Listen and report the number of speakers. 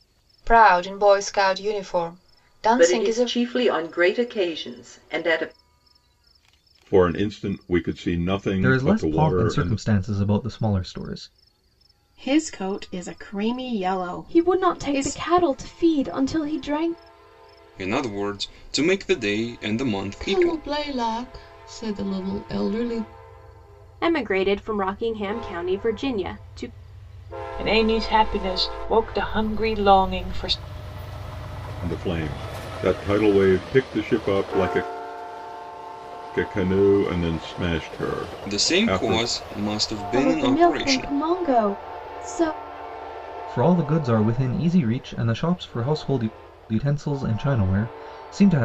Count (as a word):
ten